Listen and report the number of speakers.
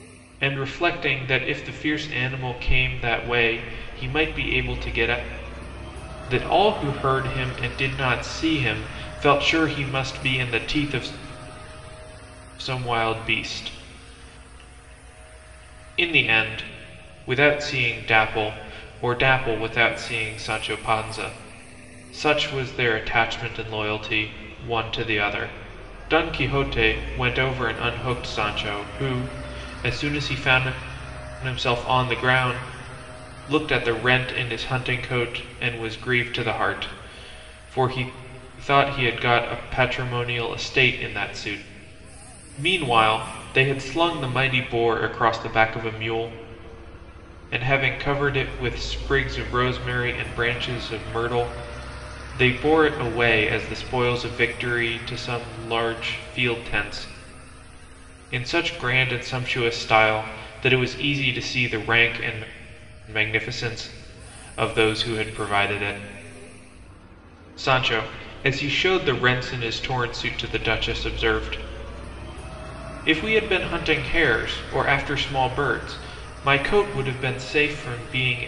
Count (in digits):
1